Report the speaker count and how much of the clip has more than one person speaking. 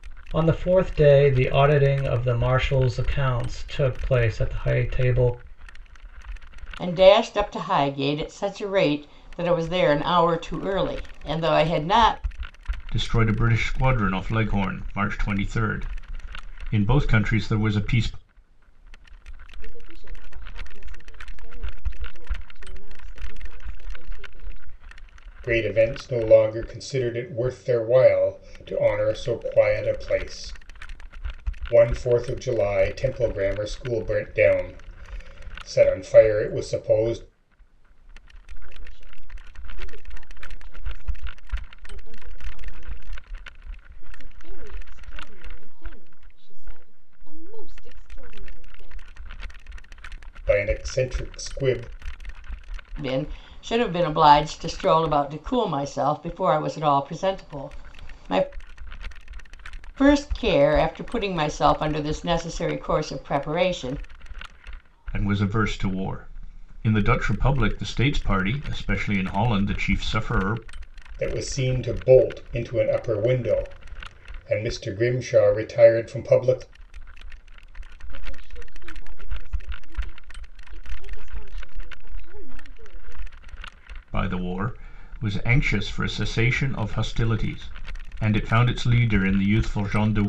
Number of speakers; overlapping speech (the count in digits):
5, no overlap